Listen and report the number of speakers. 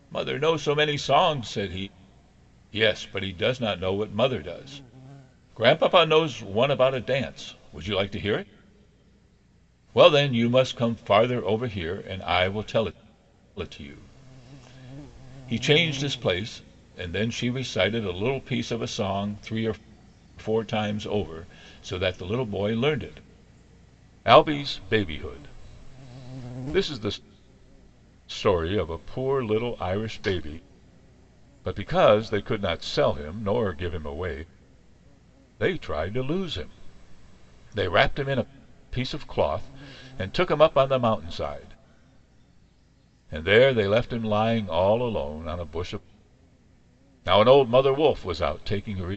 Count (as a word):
one